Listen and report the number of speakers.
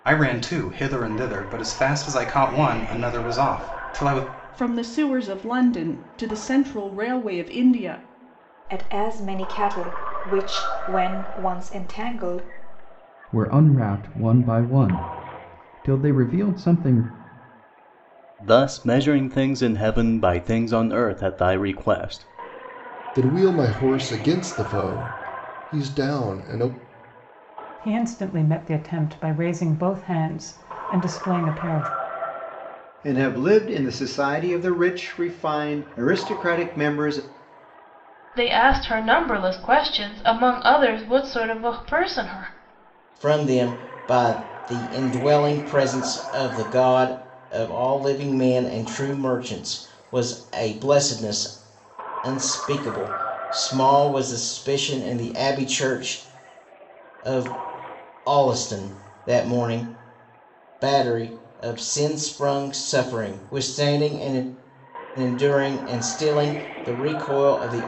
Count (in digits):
10